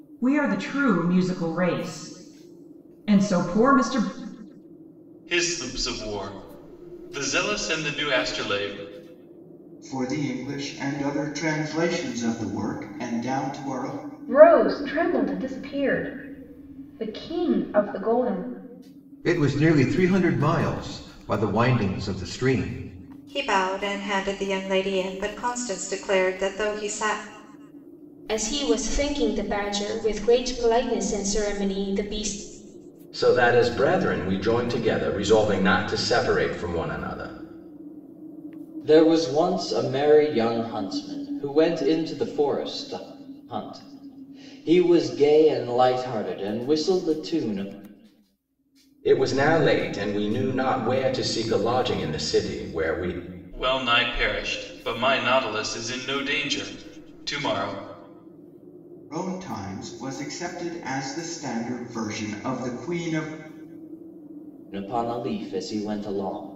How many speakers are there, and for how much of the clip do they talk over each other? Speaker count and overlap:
nine, no overlap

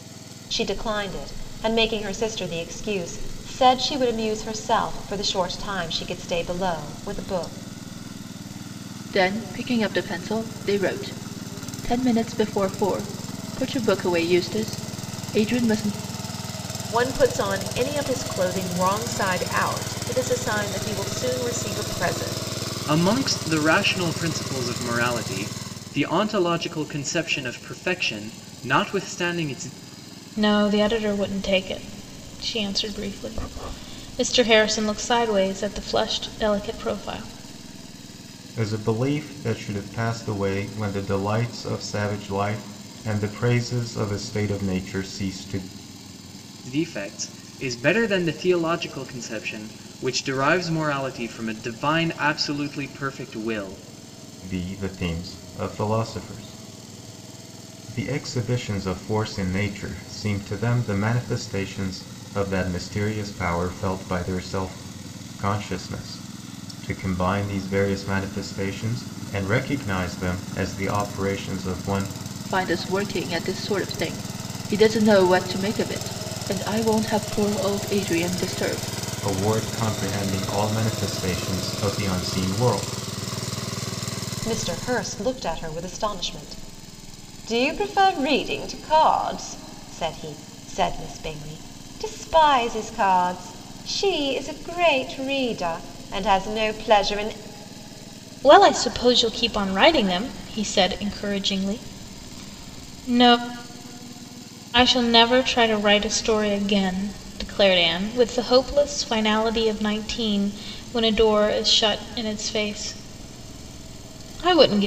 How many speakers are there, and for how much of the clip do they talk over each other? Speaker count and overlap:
six, no overlap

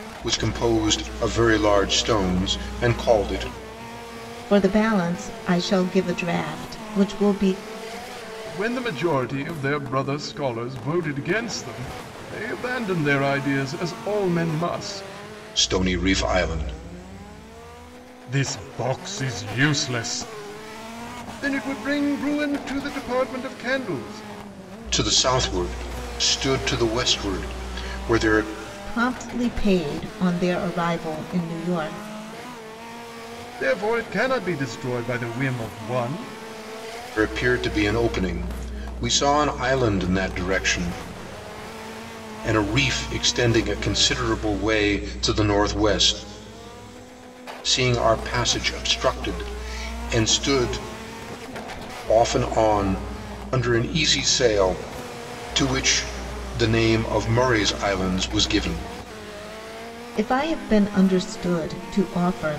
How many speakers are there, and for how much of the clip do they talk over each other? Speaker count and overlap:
three, no overlap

